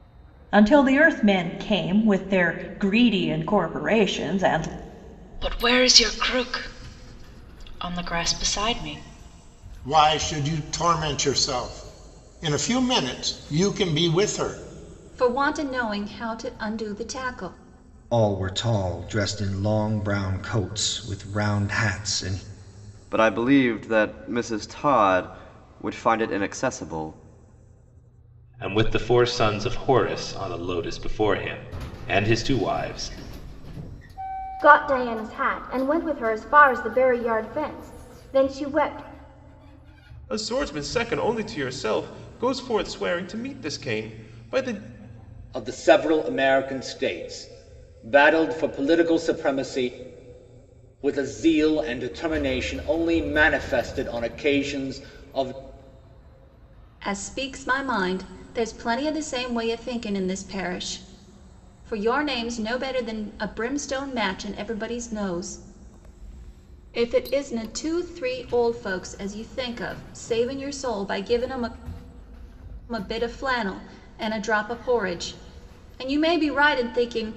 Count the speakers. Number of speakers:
10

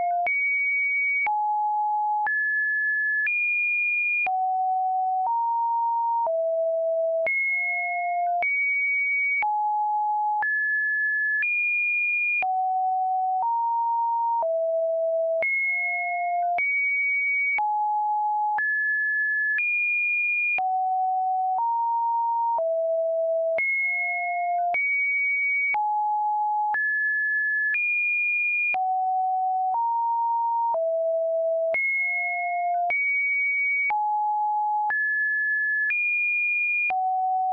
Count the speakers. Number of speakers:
0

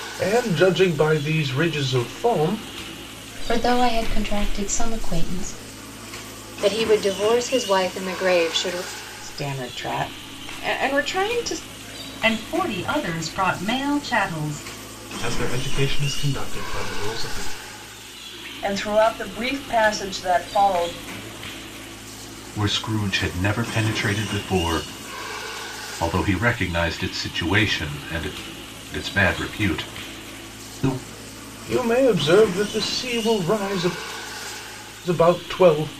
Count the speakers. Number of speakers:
8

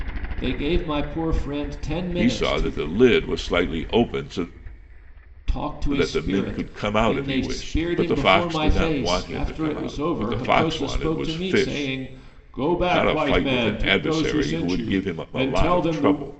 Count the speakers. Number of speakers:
2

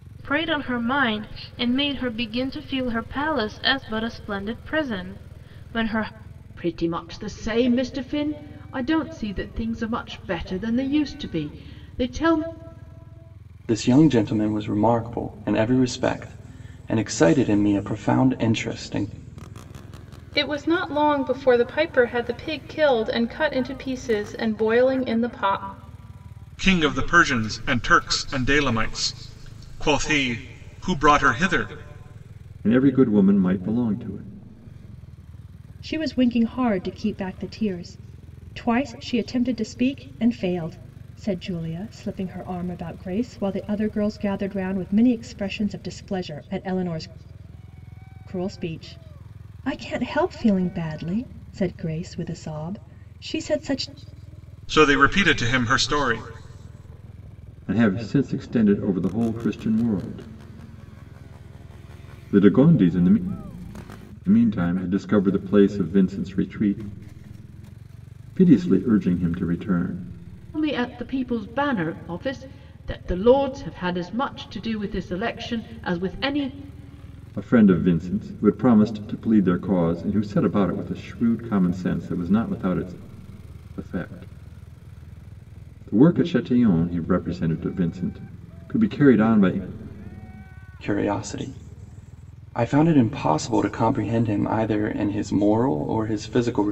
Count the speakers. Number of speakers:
7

